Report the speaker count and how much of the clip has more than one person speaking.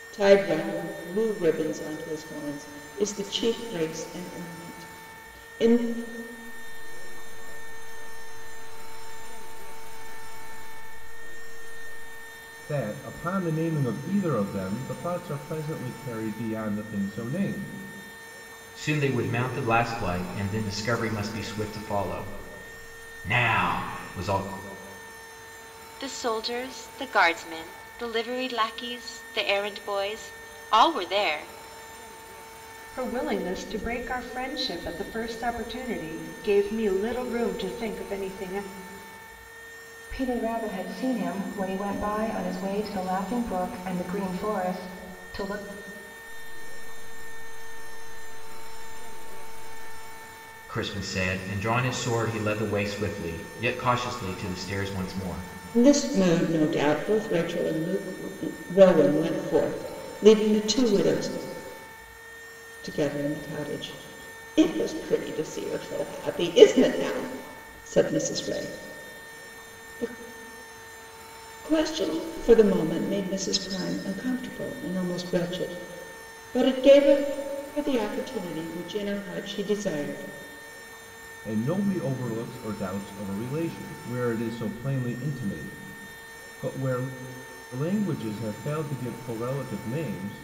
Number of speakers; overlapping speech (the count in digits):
7, no overlap